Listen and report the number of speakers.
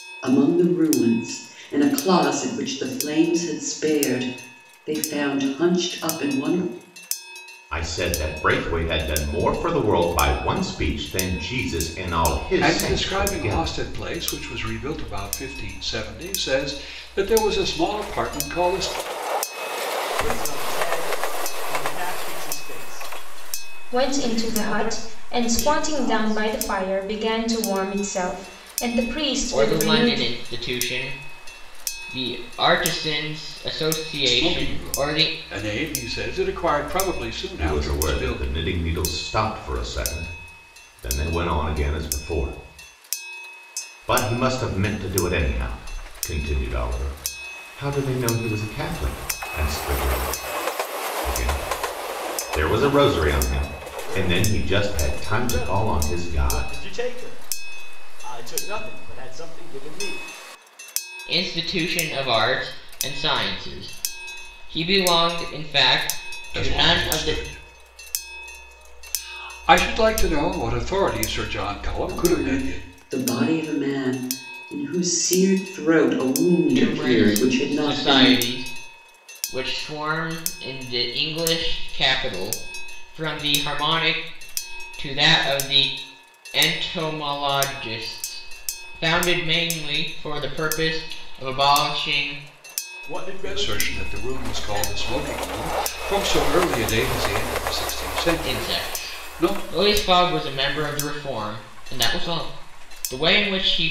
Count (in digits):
6